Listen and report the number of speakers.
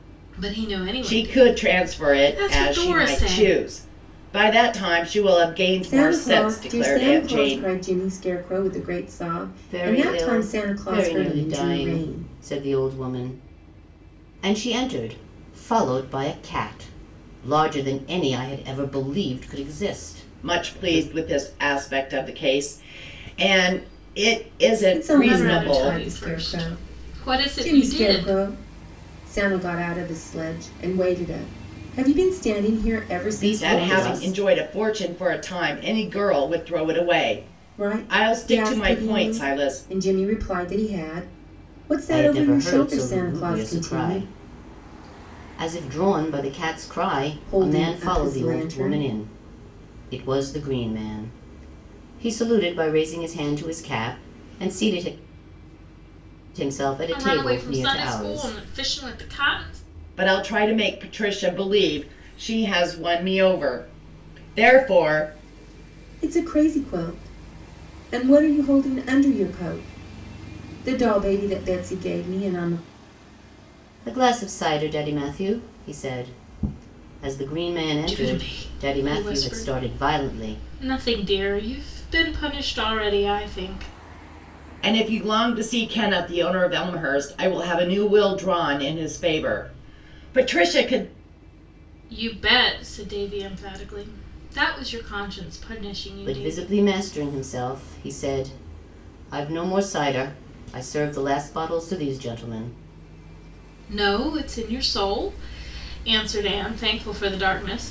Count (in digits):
4